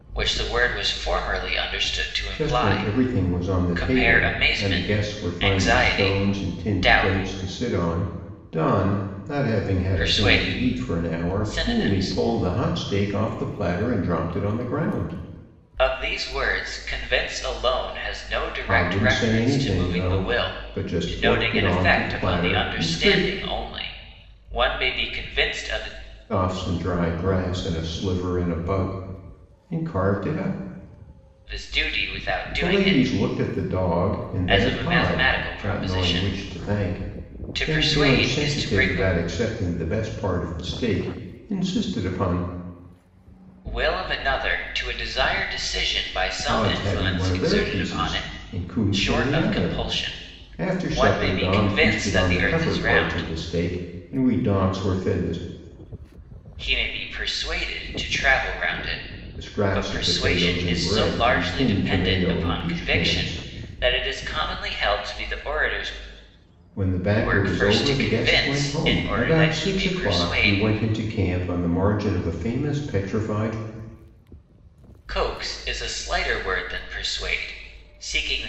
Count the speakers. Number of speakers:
2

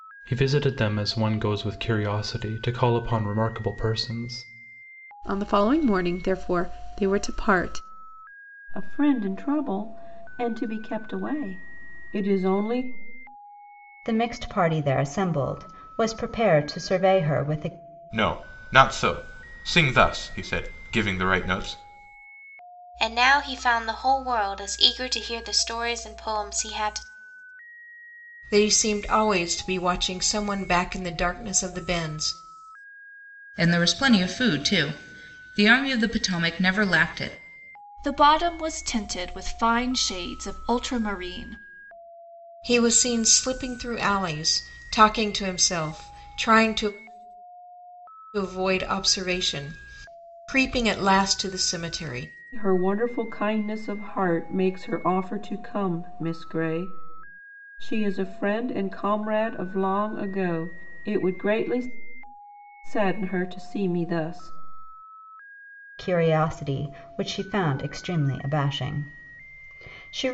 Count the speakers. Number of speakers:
9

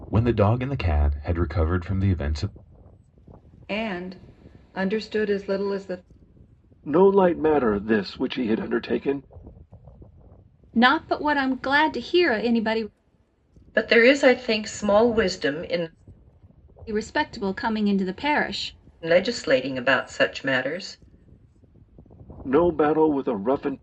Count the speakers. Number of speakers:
5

